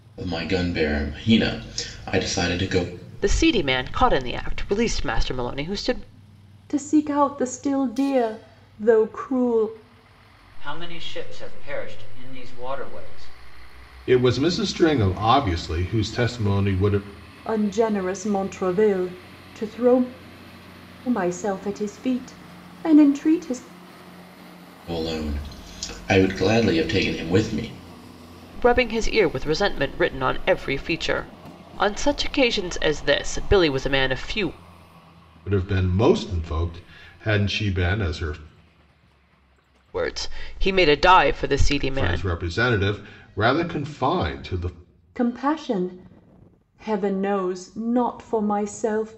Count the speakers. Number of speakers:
five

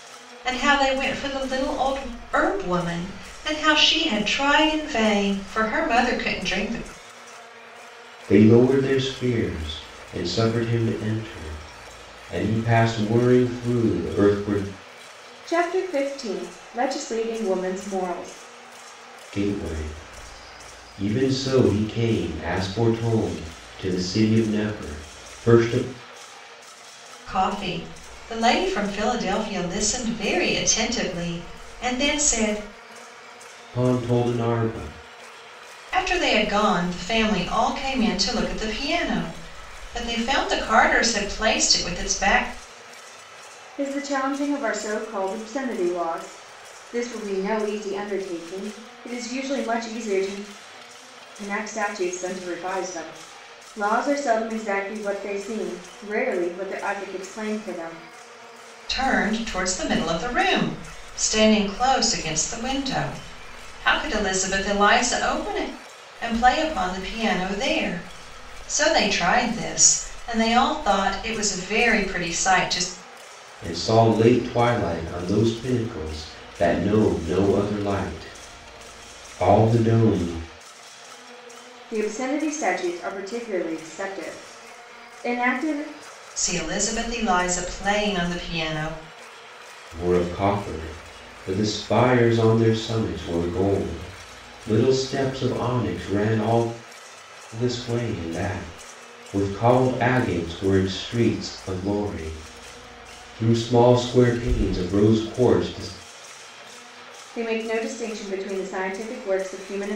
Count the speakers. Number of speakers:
three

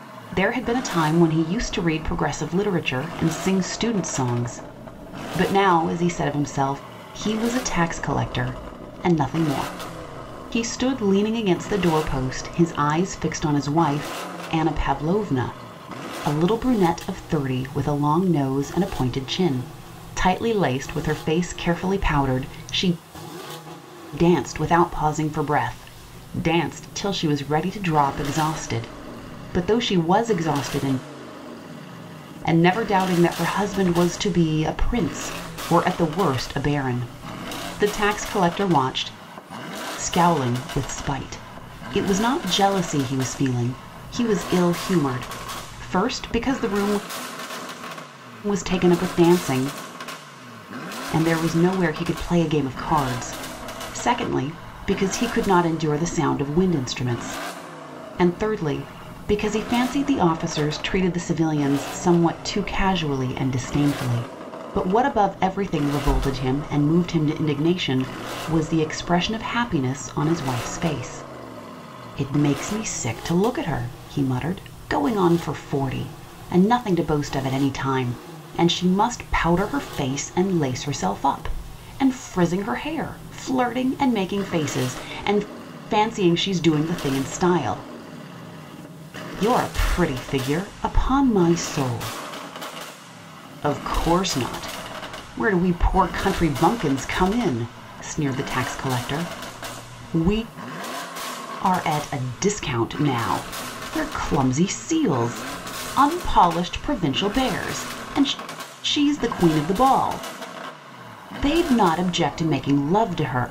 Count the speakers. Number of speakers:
one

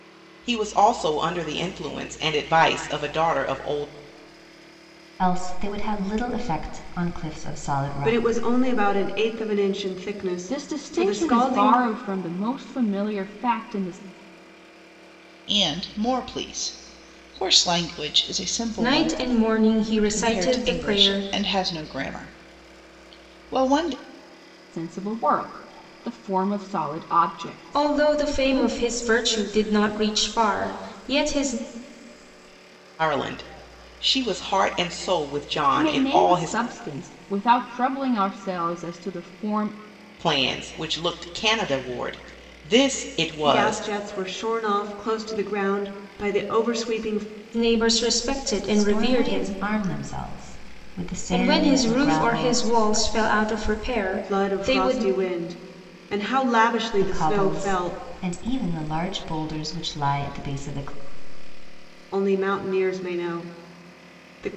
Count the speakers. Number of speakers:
six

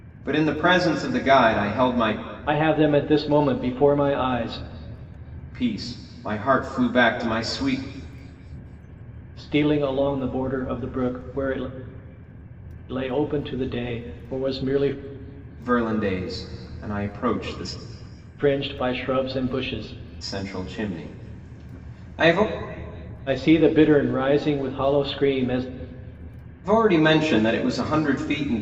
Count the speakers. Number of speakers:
two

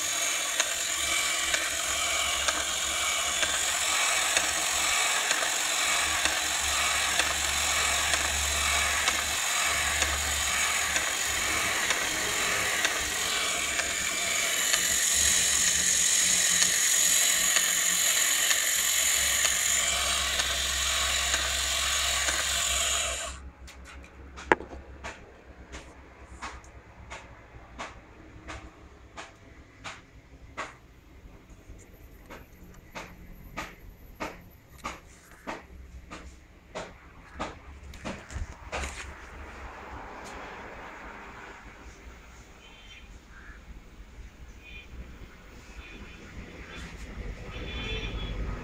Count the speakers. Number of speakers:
zero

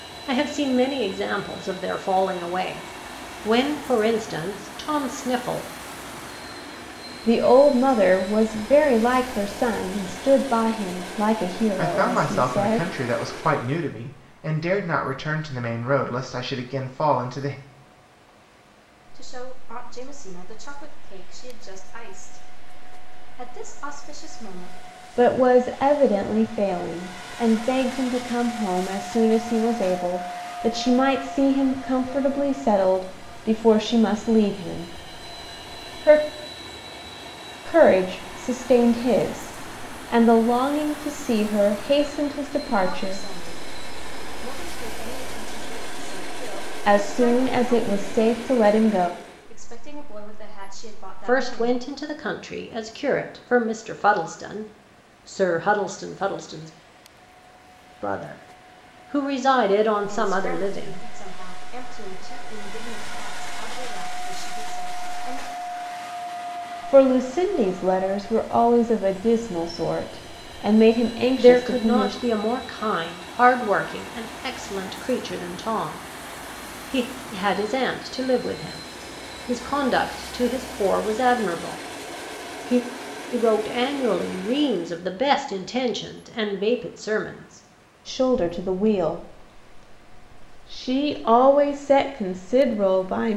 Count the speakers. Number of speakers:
four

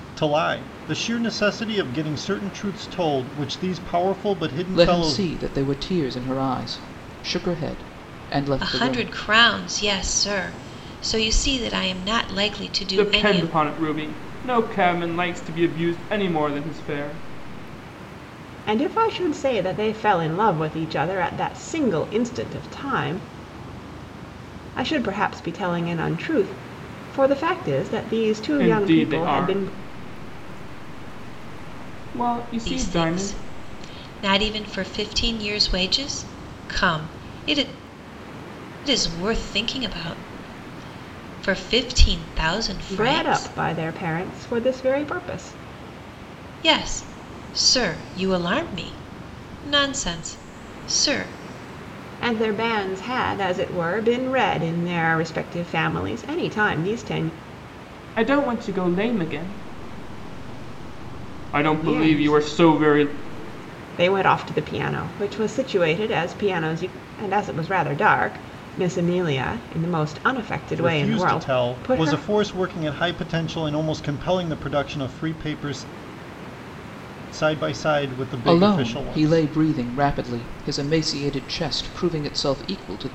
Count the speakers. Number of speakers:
five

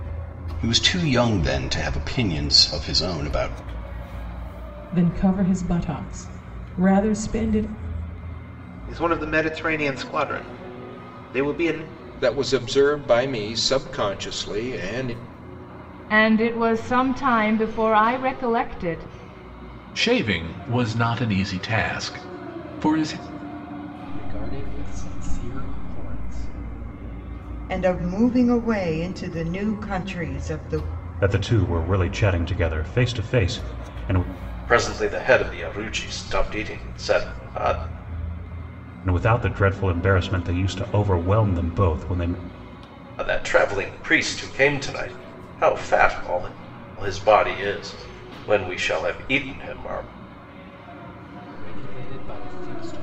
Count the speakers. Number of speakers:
ten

